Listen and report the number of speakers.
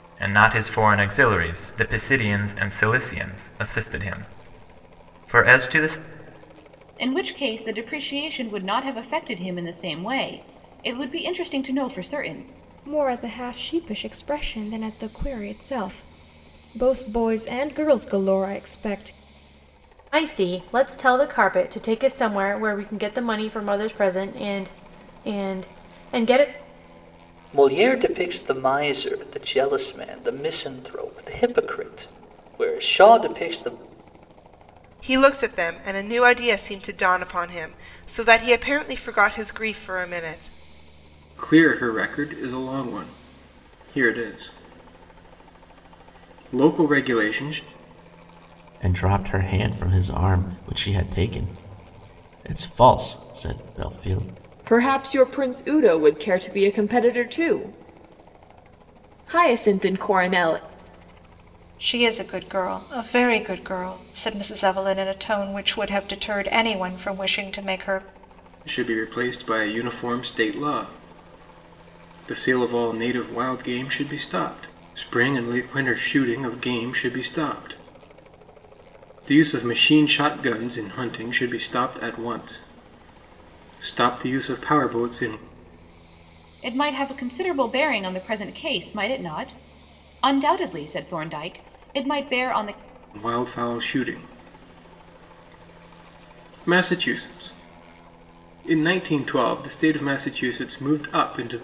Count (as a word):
ten